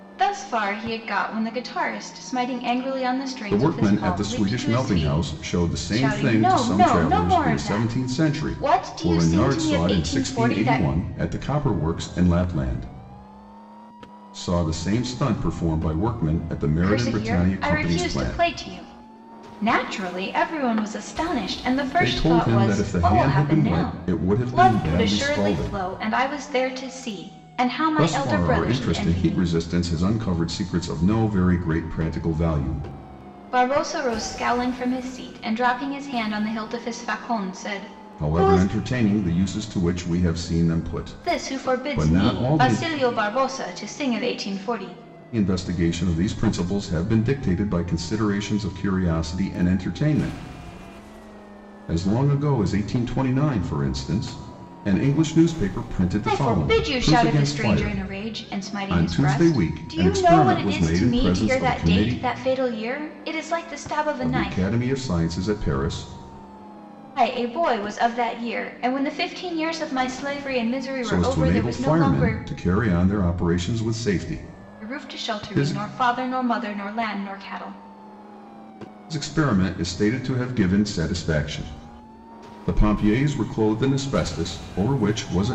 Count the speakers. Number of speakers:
2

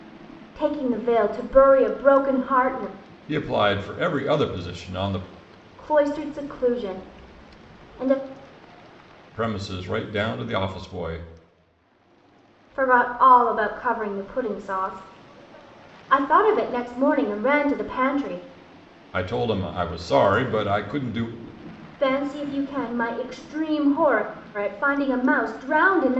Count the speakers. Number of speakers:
2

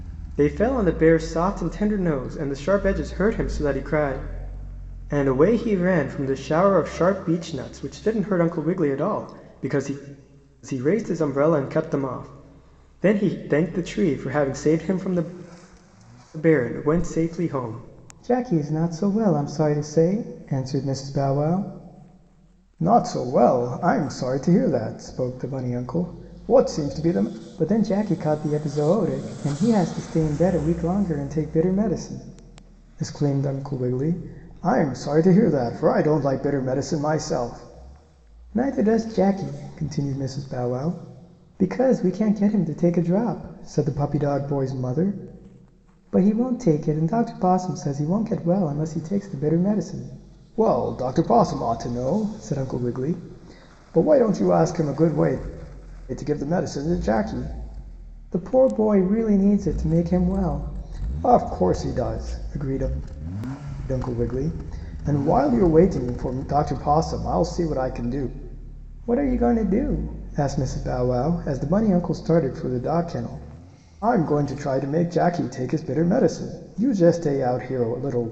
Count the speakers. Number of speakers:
1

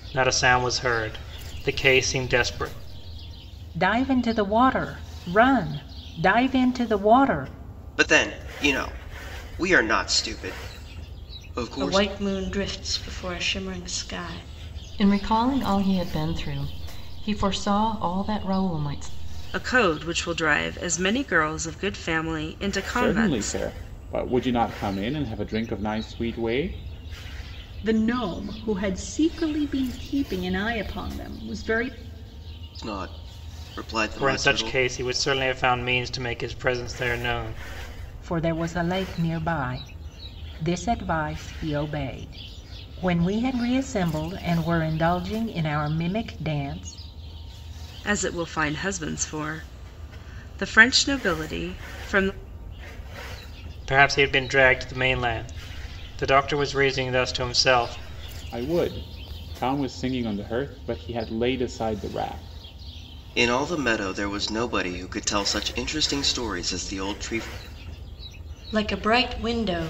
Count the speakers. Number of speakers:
8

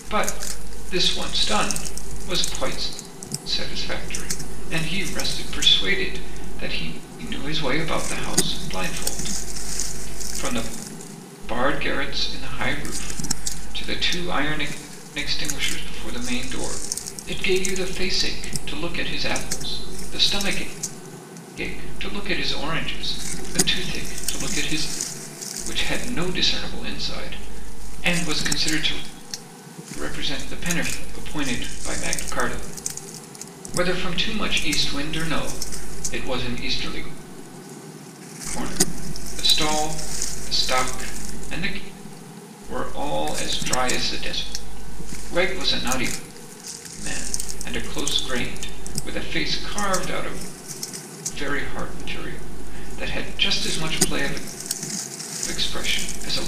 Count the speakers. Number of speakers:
1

